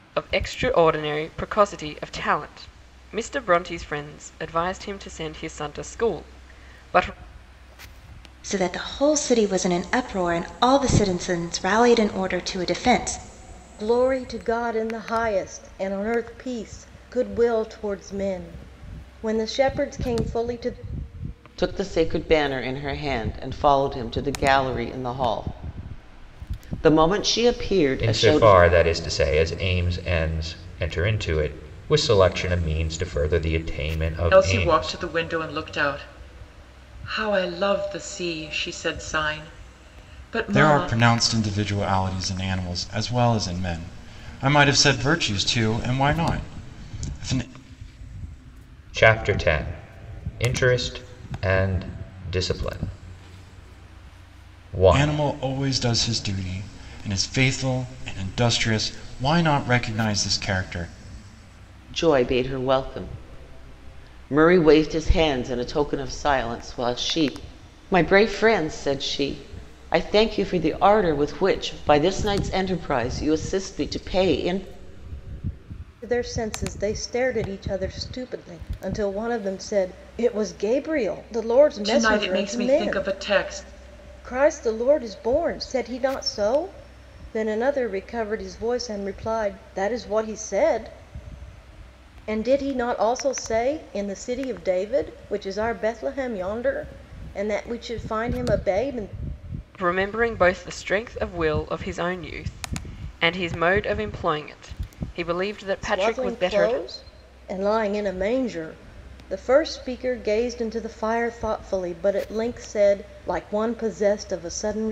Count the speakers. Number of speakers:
7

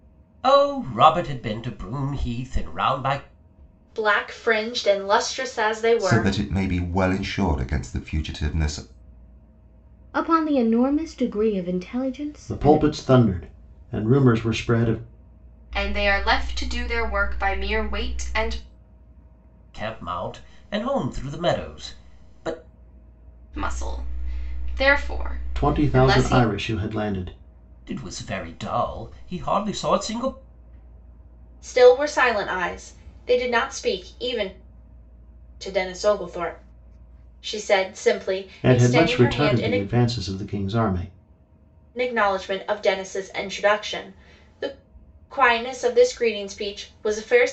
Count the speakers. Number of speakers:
6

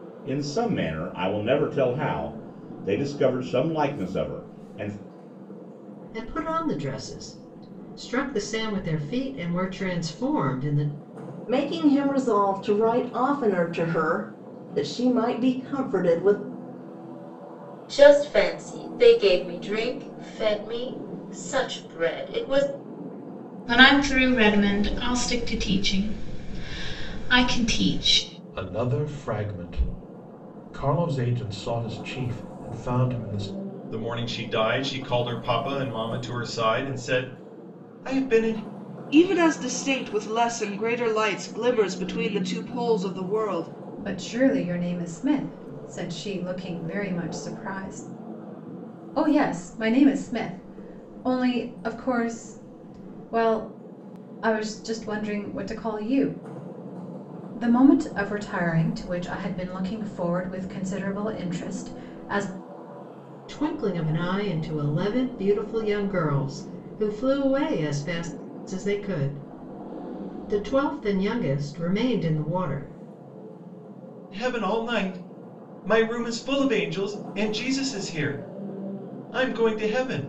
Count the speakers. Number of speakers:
9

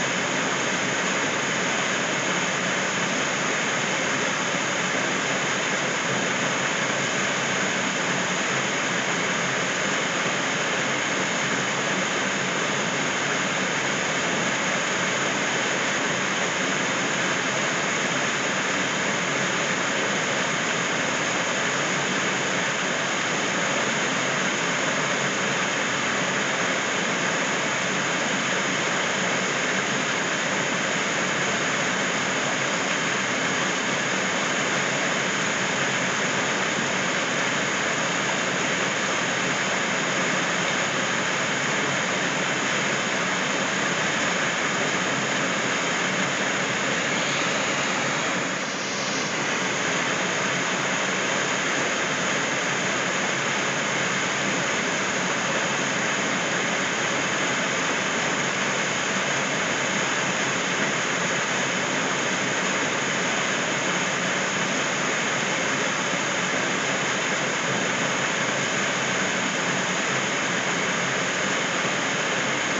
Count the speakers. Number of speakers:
0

